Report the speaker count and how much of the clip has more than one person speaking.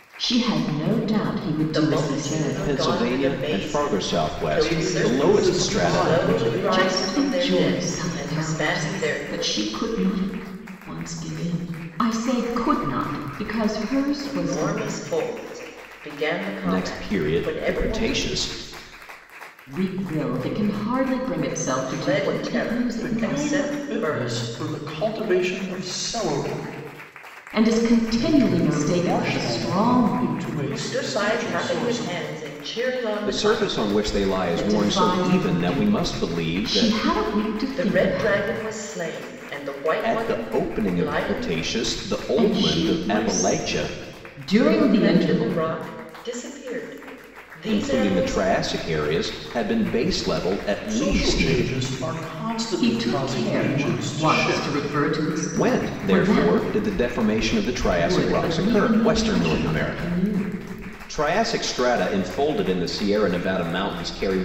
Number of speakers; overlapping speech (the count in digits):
4, about 50%